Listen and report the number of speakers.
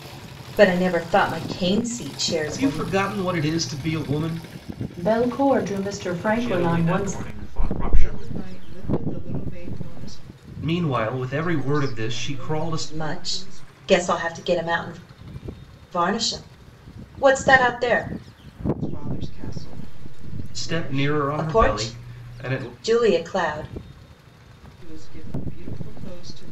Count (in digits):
5